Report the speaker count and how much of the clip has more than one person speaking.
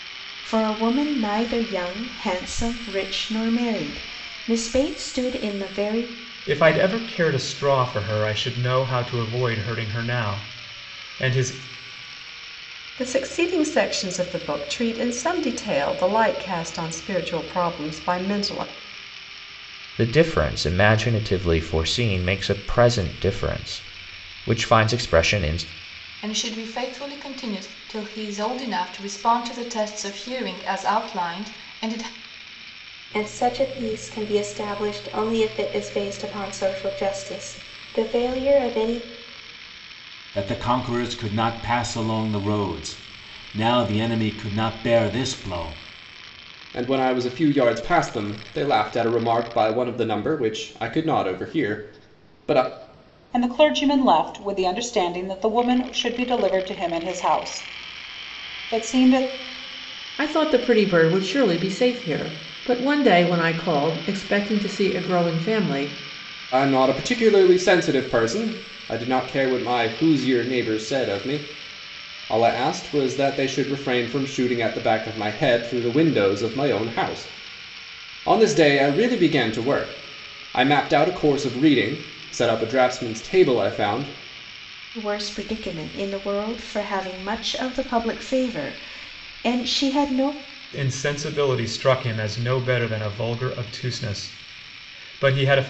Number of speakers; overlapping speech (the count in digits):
10, no overlap